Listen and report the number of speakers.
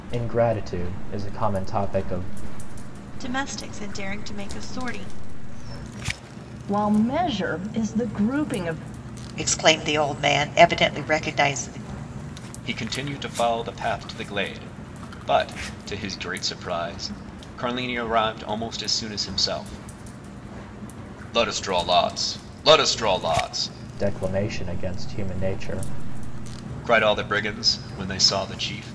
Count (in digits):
5